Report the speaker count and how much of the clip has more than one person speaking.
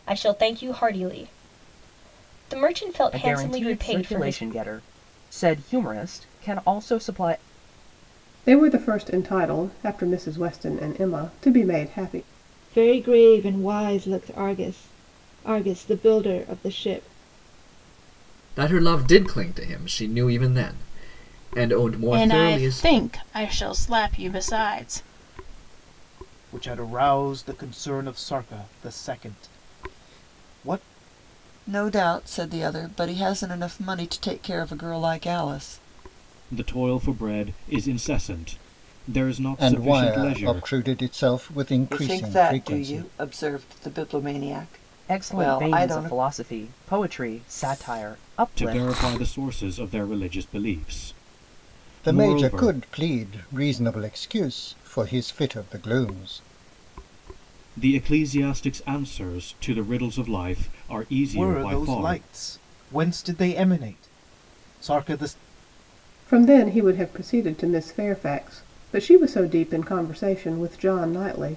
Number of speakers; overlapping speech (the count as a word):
ten, about 11%